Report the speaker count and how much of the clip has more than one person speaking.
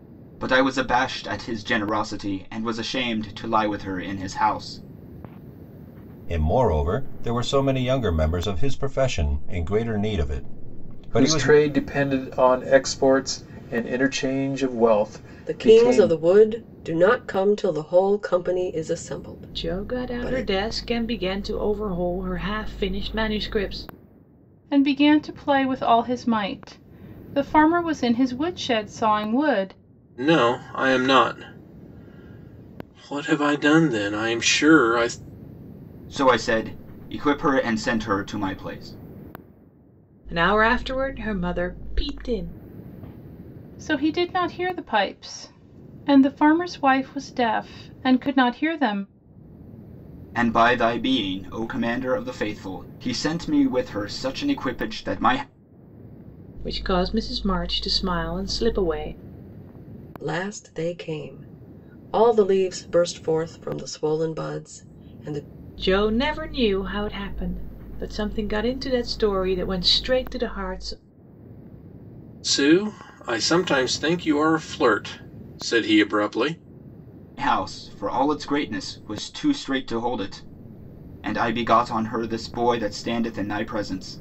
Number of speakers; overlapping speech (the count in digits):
7, about 3%